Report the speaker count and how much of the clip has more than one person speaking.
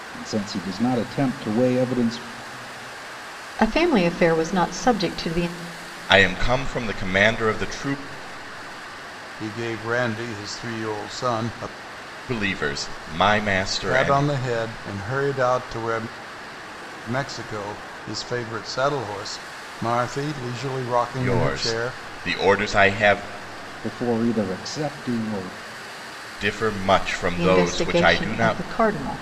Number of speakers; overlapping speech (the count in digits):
4, about 9%